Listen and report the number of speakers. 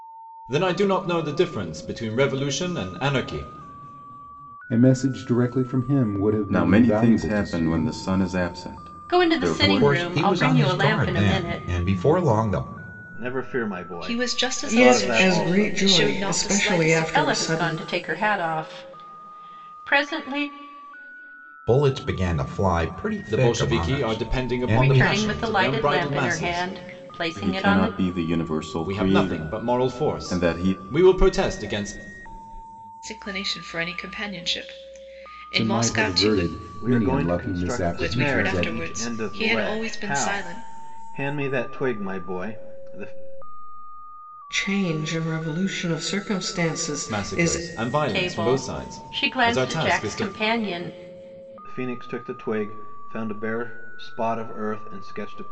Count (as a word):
eight